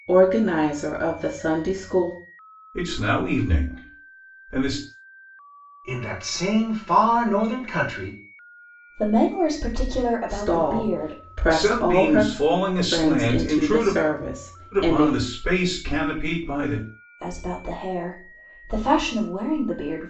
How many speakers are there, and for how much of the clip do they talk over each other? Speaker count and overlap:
four, about 17%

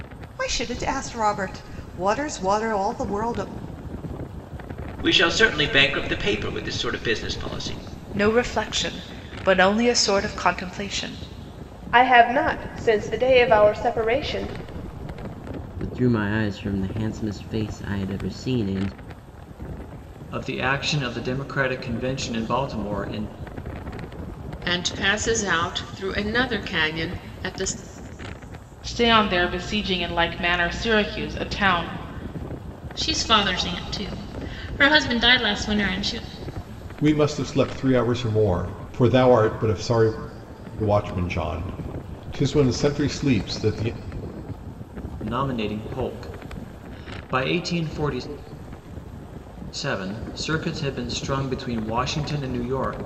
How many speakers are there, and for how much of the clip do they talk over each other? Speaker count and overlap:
ten, no overlap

